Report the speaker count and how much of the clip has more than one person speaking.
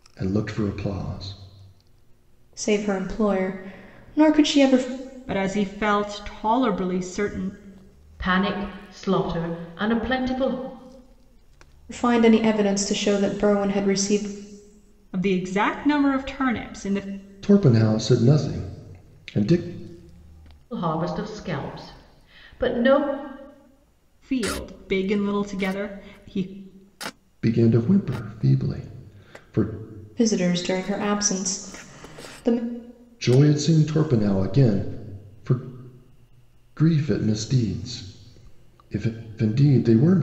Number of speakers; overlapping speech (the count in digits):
4, no overlap